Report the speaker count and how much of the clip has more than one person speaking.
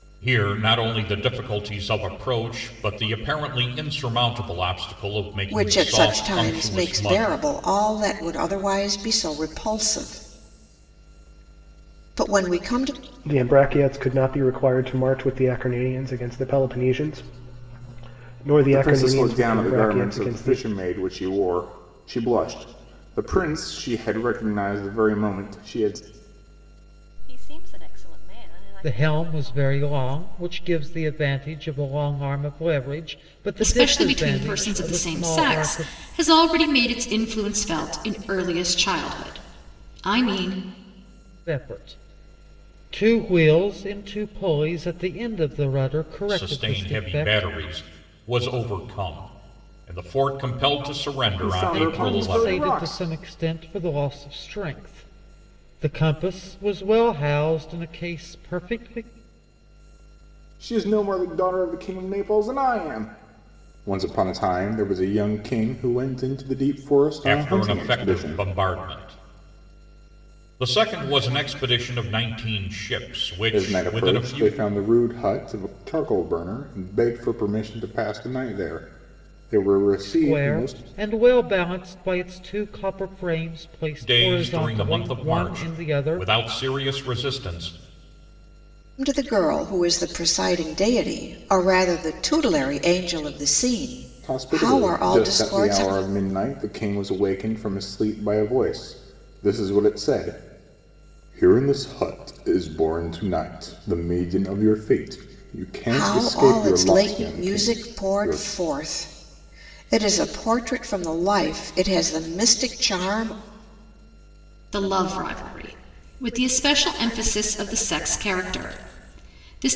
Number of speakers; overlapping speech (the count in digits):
7, about 17%